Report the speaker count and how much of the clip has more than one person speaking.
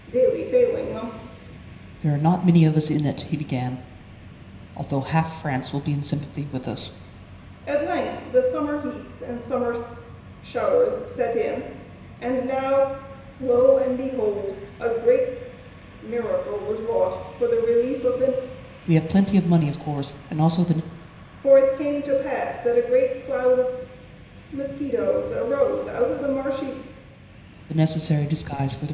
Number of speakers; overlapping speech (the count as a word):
two, no overlap